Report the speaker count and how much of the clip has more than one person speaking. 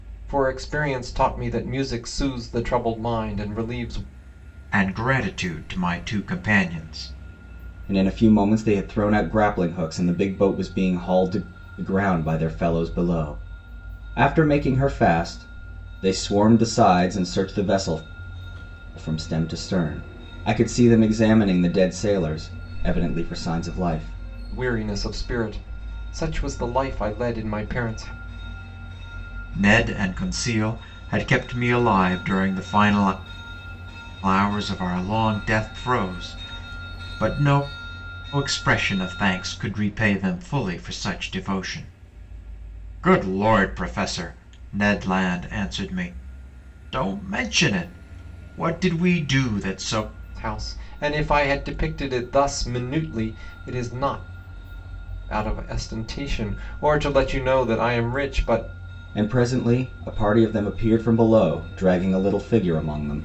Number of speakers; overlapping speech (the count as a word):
three, no overlap